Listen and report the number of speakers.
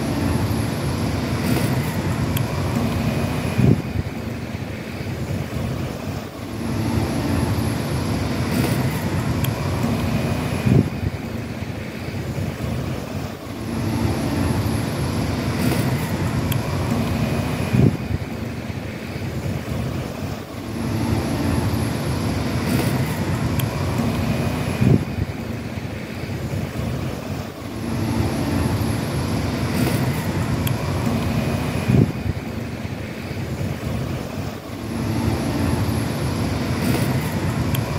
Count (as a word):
zero